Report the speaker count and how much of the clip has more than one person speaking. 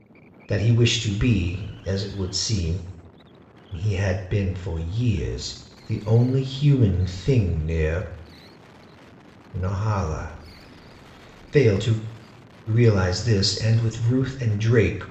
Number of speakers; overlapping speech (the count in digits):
1, no overlap